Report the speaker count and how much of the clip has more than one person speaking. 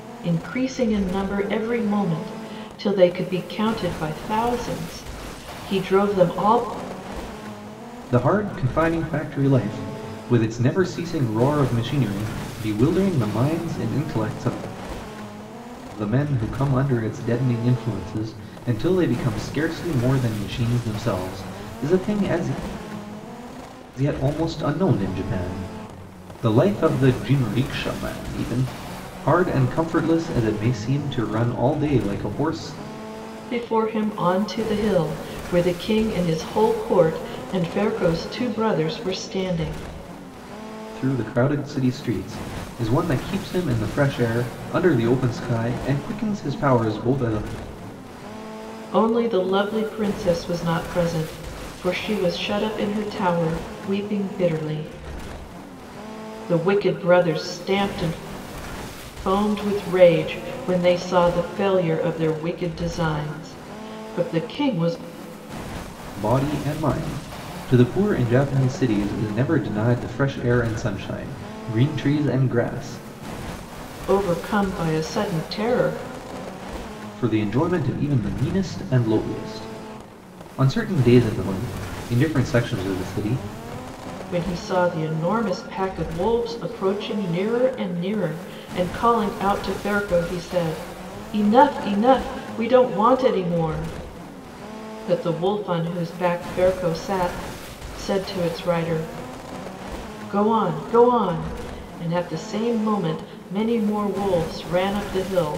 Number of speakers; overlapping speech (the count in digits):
2, no overlap